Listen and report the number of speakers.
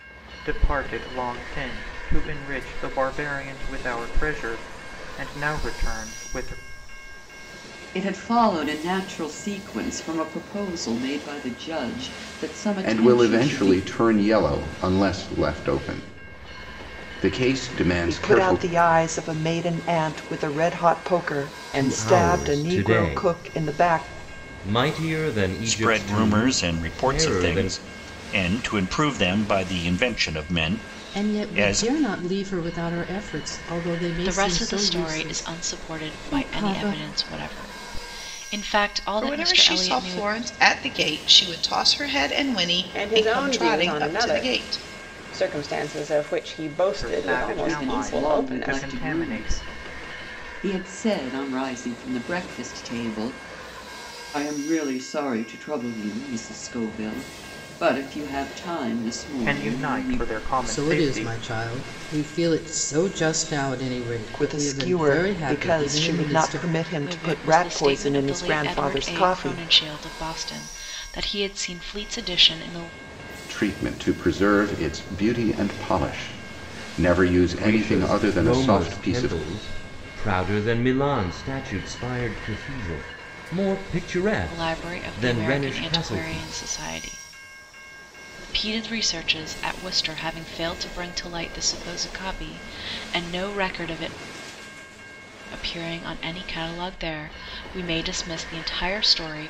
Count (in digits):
10